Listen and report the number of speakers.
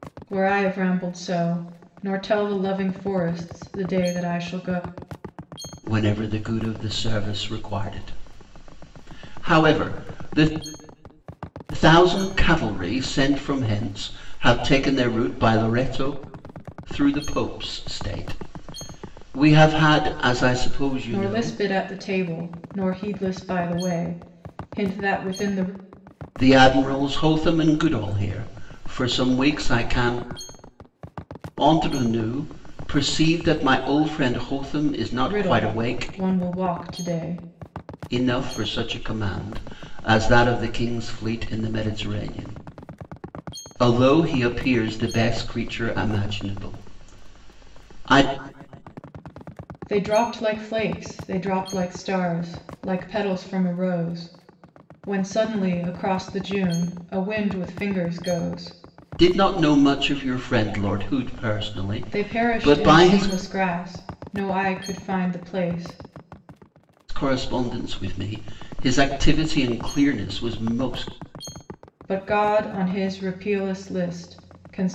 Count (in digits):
2